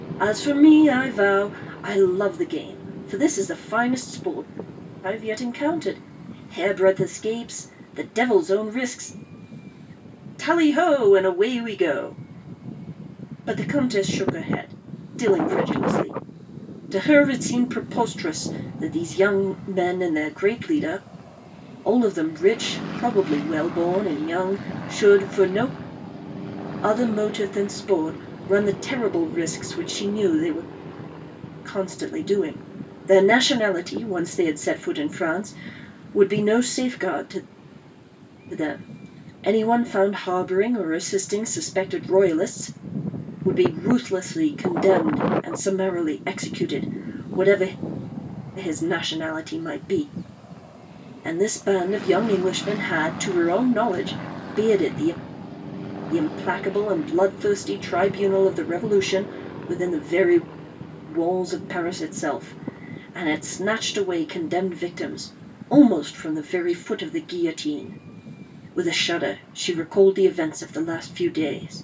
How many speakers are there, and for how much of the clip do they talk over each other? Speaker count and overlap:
1, no overlap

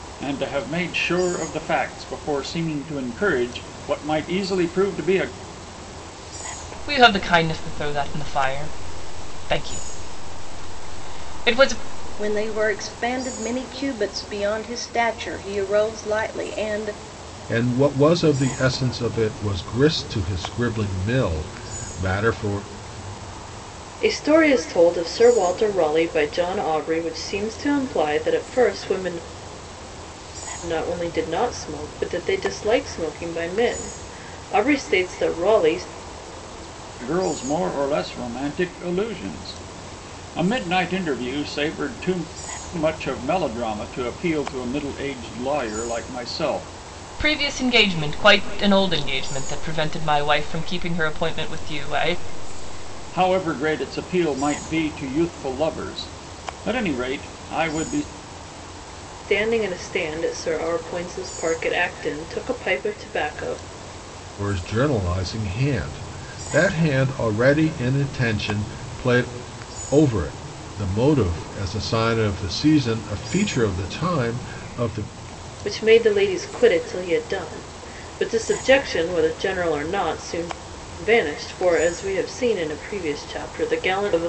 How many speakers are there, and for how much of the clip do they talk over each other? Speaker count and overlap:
5, no overlap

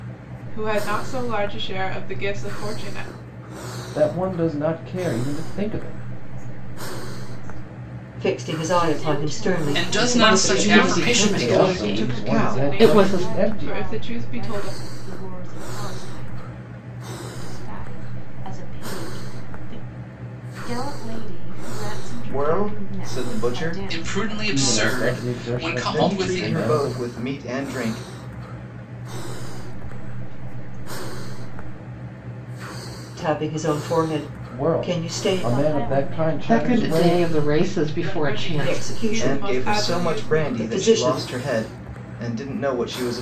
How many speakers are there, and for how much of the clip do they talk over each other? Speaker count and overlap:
8, about 45%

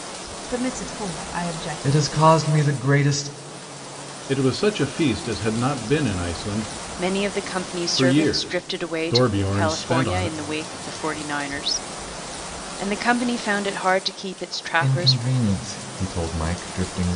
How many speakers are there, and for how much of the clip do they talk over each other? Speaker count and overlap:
4, about 18%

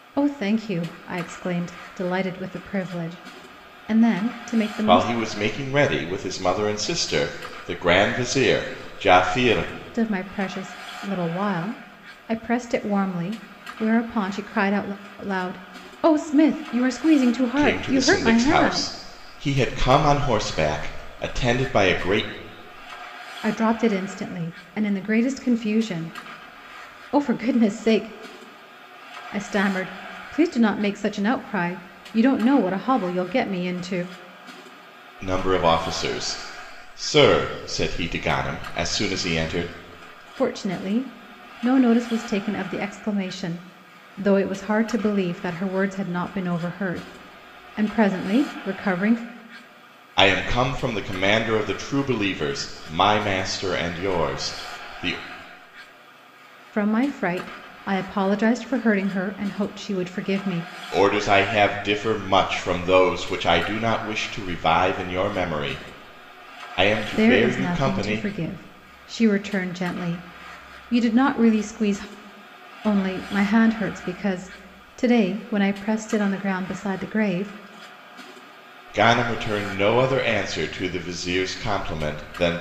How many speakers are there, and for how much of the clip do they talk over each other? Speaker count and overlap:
2, about 4%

